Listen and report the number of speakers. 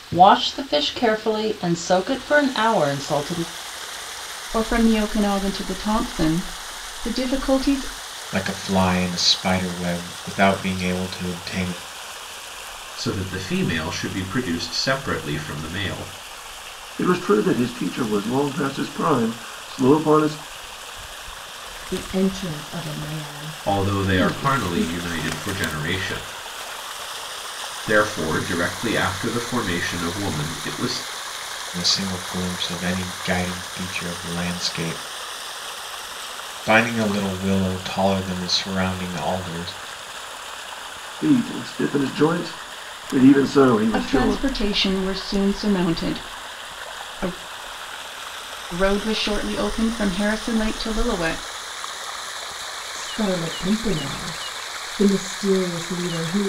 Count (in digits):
6